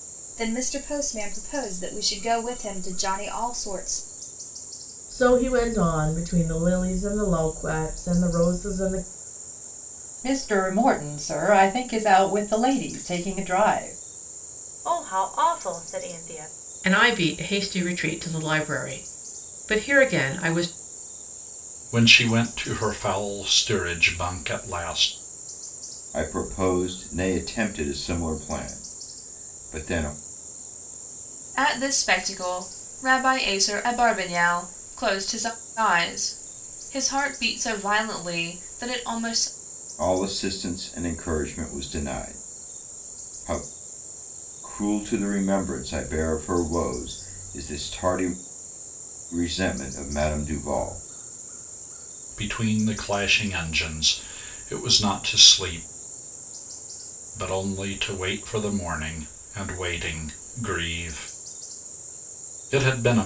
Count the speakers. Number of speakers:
8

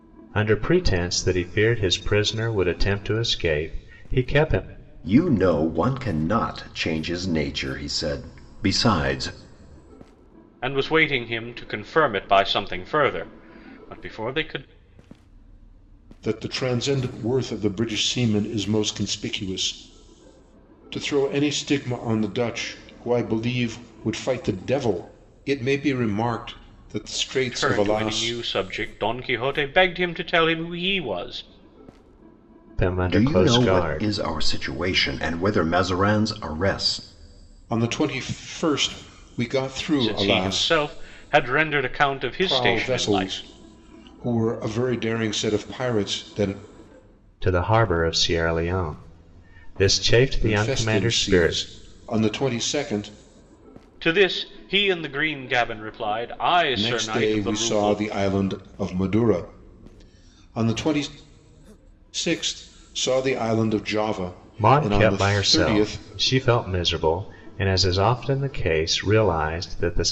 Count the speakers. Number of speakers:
4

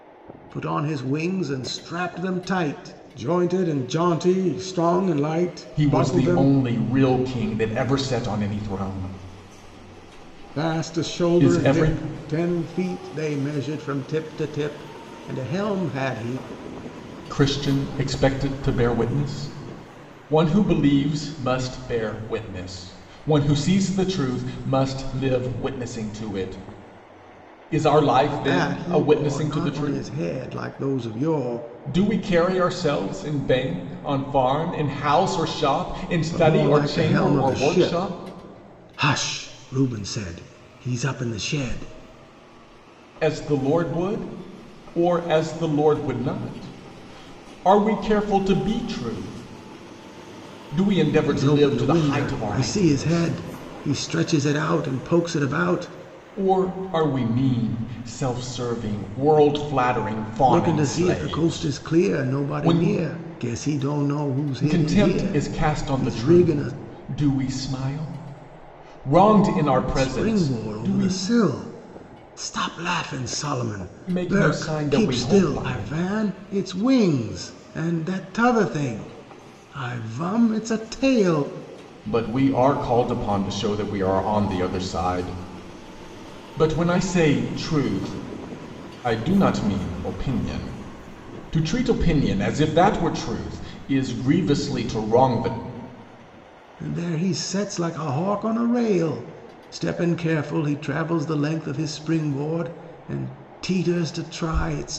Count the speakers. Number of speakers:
2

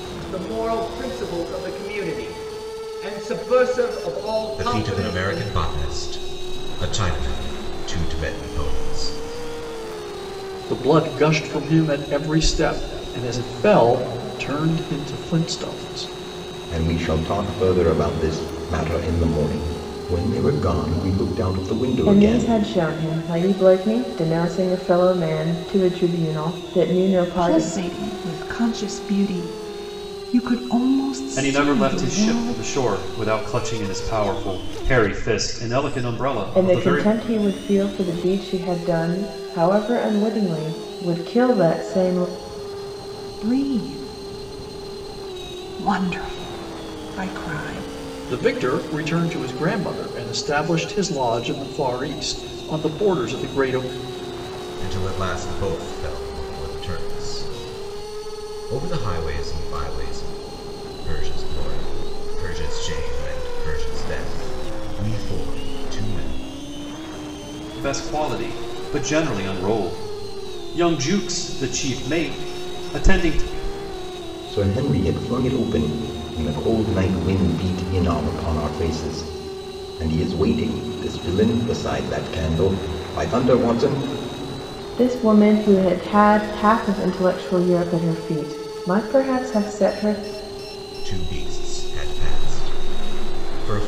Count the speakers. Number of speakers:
7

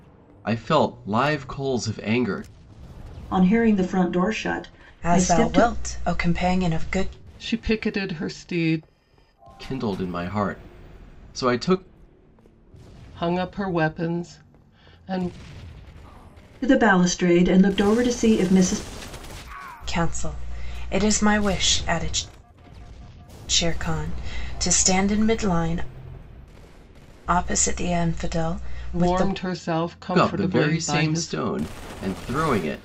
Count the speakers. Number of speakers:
4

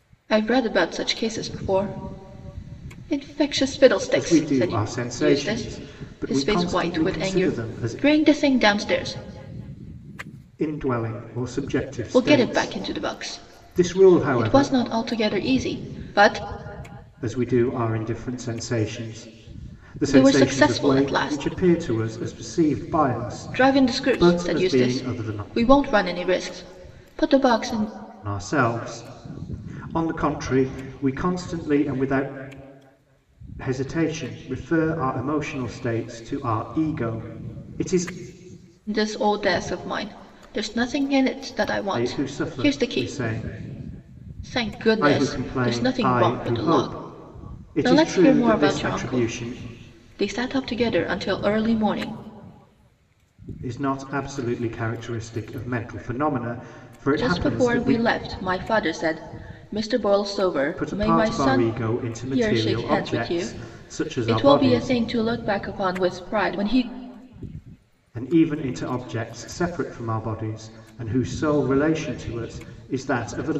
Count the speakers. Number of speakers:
2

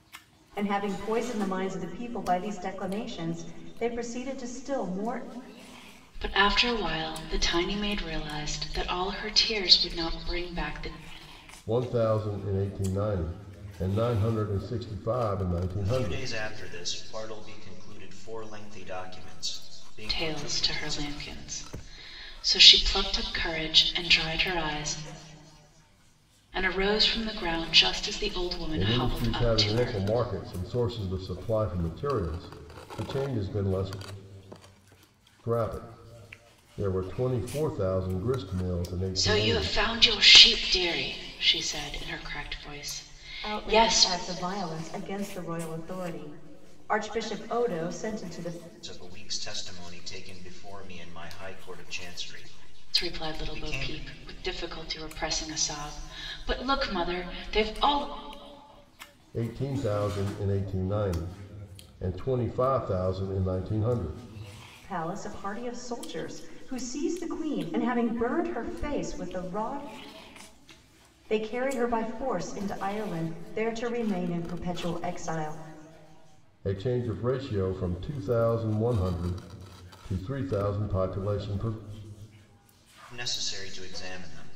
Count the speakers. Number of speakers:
4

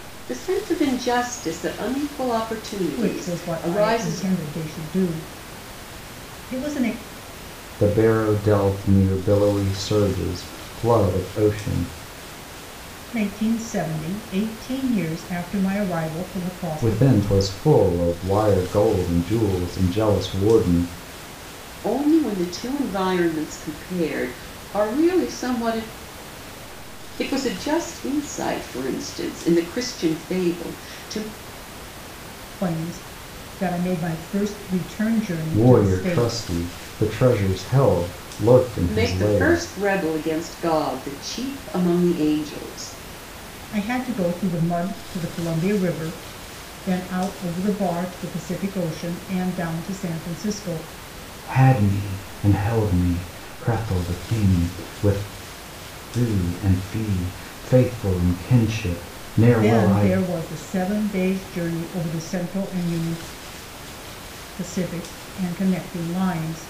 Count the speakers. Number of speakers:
3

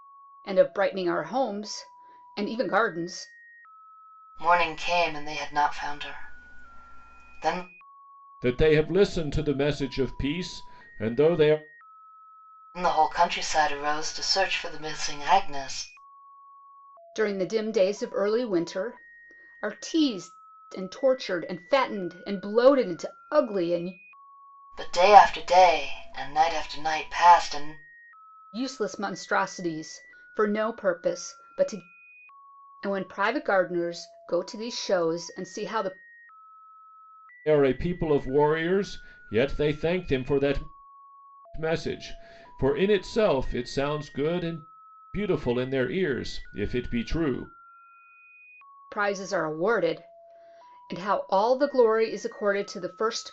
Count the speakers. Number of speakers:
3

